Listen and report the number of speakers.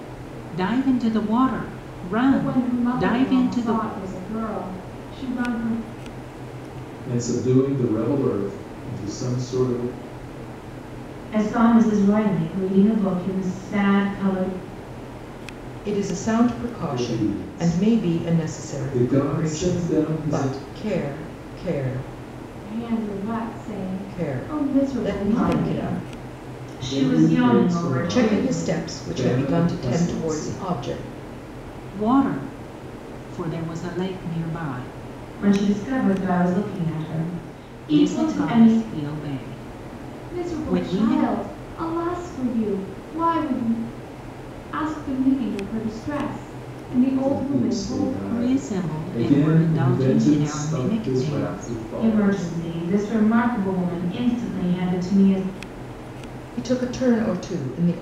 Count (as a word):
five